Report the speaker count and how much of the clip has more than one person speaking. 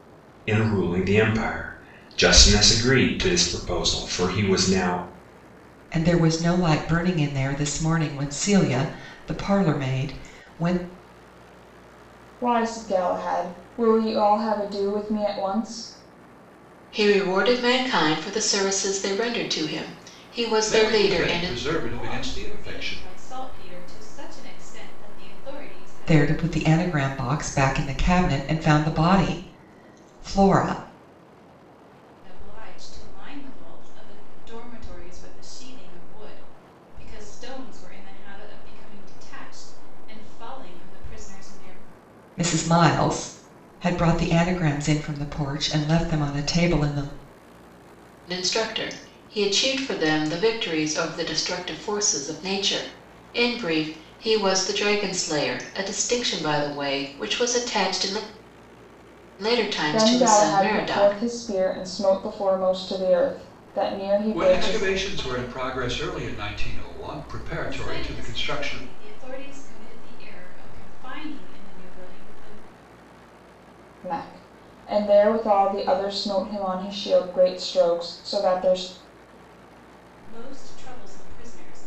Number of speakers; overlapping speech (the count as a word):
six, about 7%